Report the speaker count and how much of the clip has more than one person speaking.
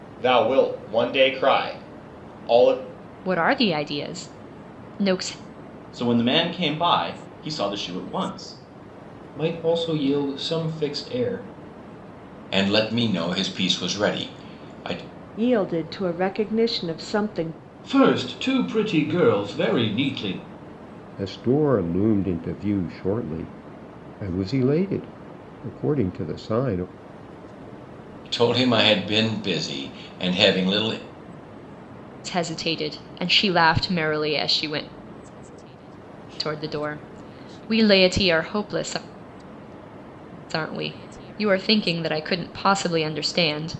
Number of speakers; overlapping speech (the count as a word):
eight, no overlap